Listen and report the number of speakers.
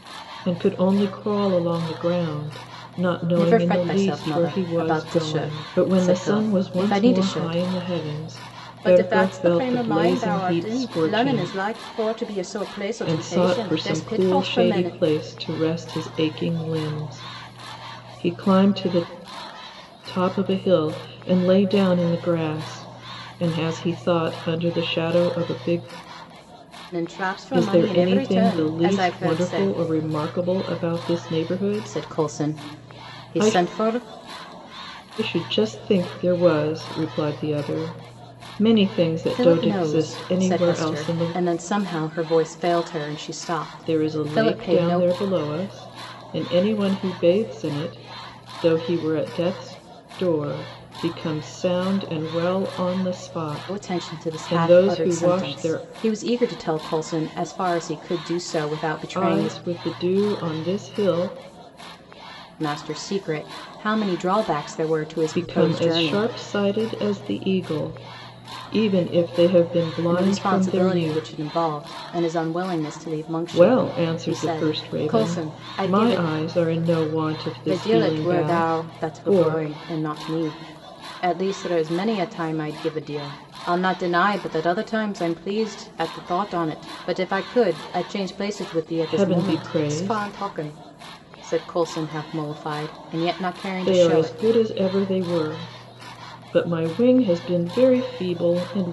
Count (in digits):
2